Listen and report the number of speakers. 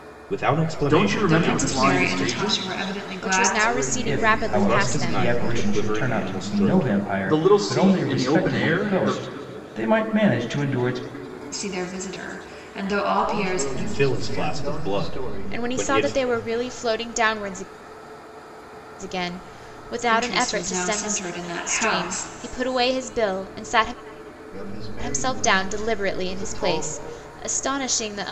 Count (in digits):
6